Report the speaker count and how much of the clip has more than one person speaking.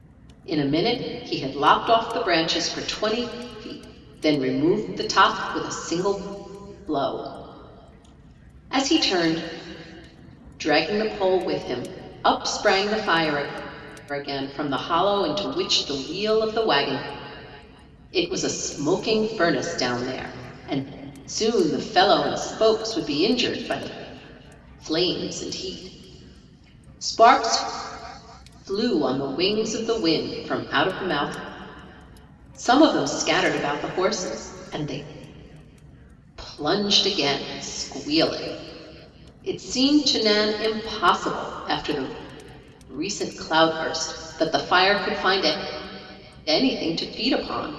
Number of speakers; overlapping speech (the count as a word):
one, no overlap